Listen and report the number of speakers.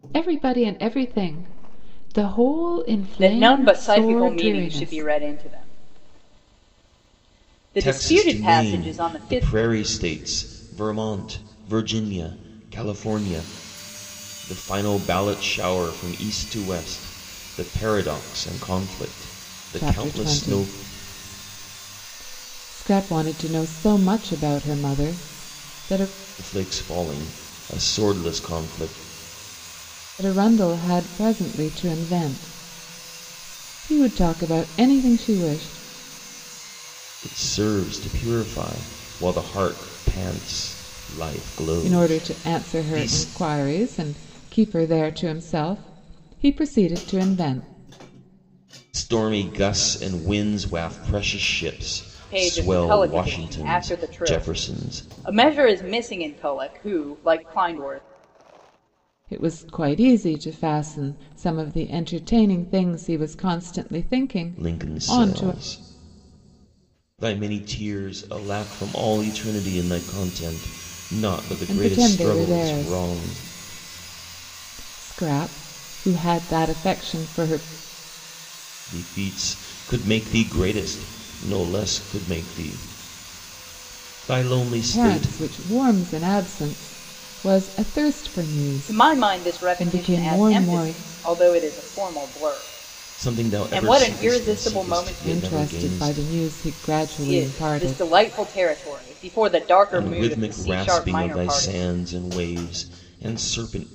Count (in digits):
3